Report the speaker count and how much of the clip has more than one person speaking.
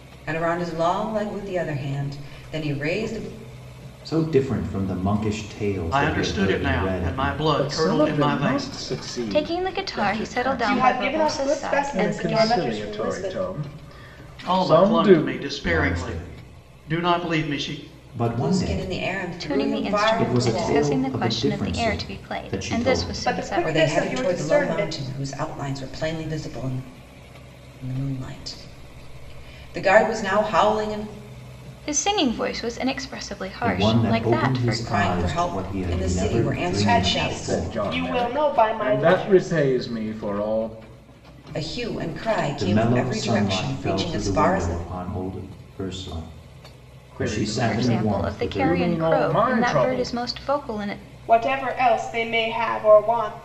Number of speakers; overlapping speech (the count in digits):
6, about 52%